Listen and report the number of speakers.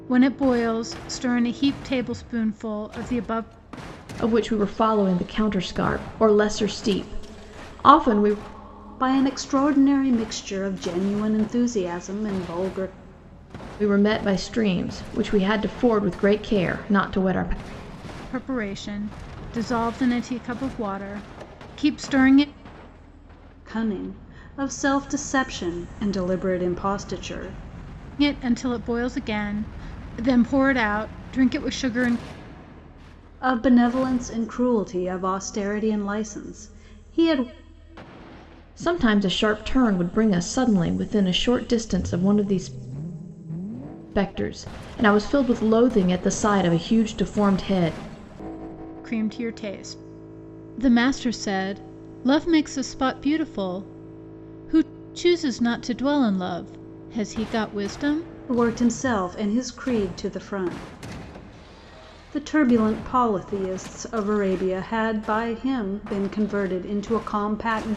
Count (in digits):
3